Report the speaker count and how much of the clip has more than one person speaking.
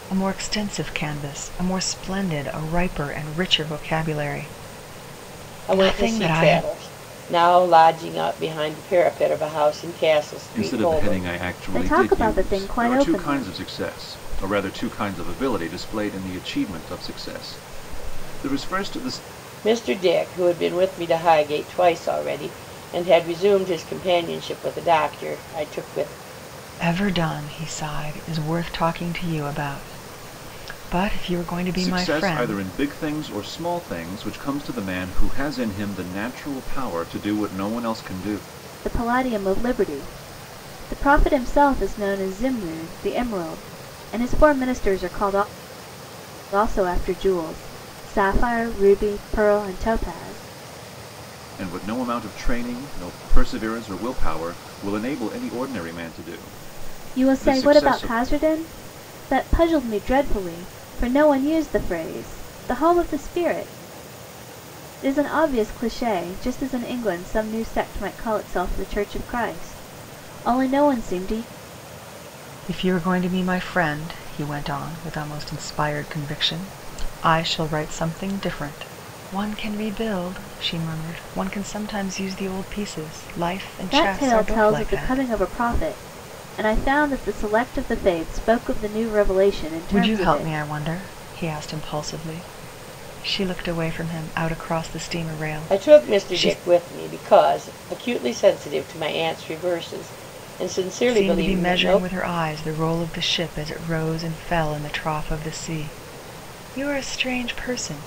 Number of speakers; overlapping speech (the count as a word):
four, about 9%